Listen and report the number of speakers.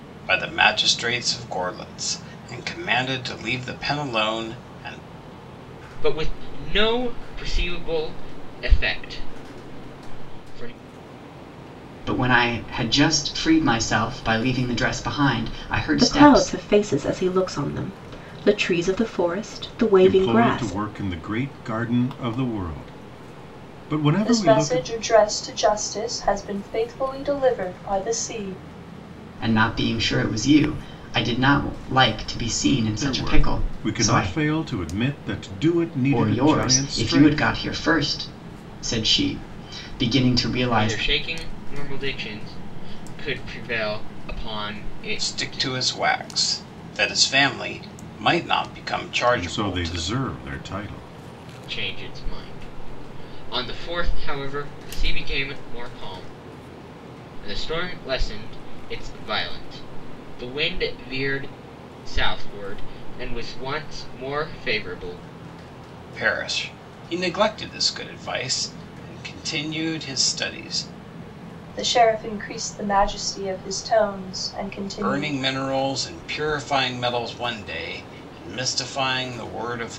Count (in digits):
6